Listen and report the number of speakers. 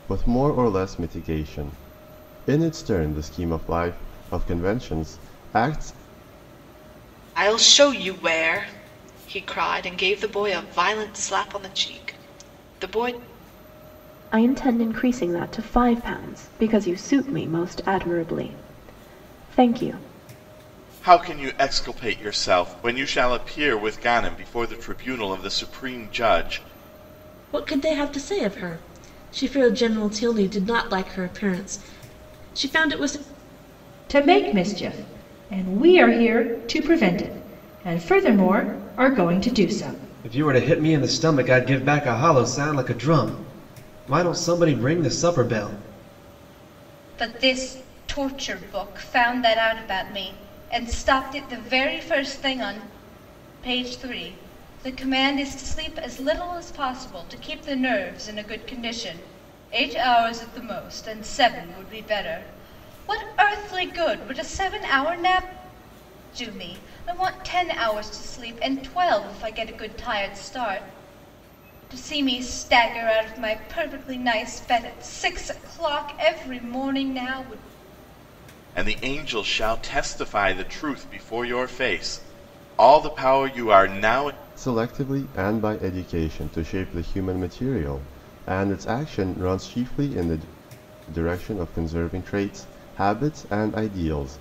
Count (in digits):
8